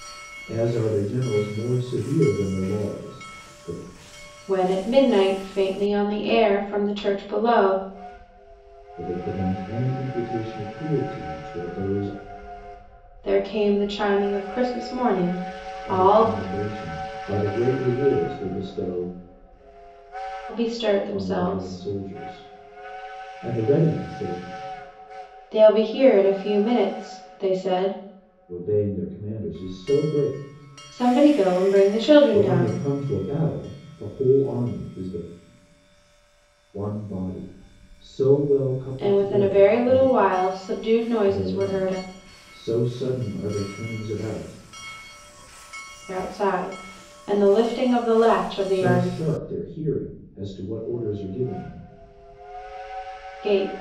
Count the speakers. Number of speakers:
two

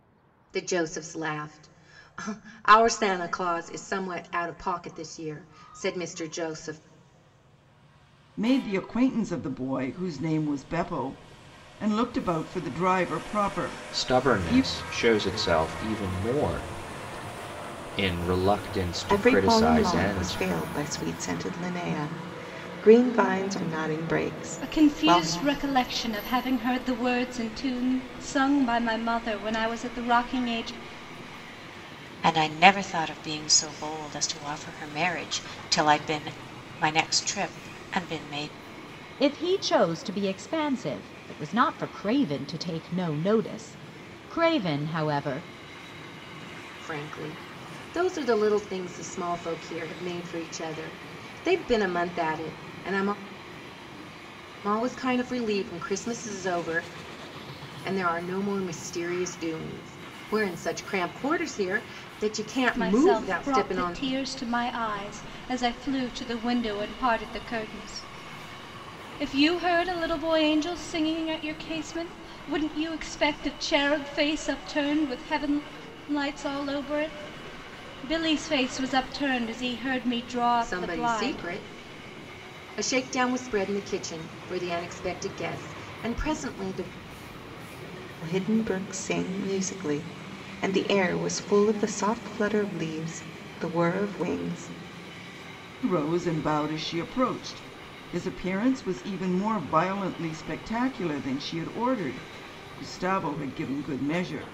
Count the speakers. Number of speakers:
seven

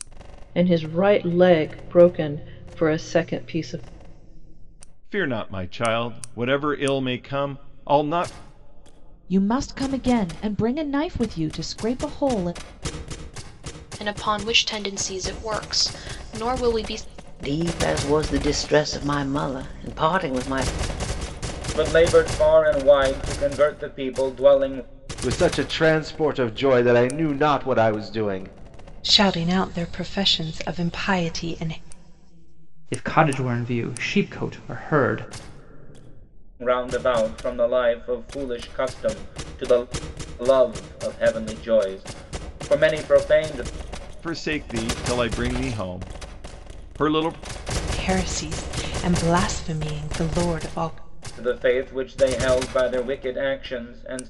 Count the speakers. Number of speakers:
nine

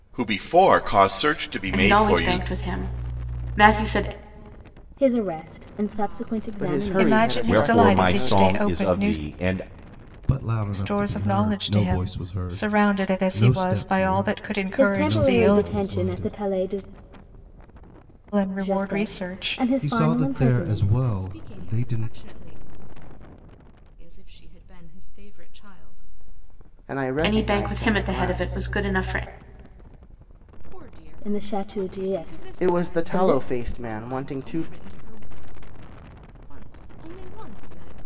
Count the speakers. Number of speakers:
eight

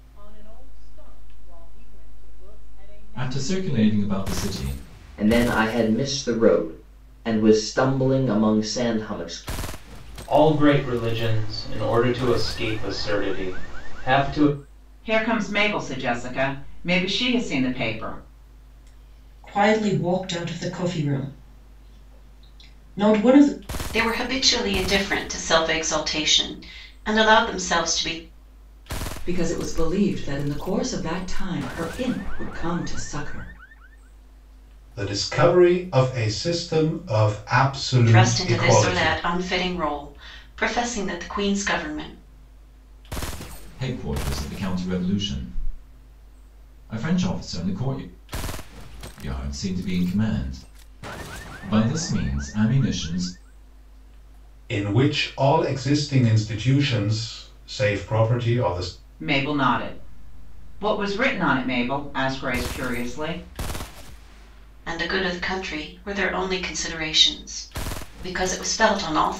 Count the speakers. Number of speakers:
nine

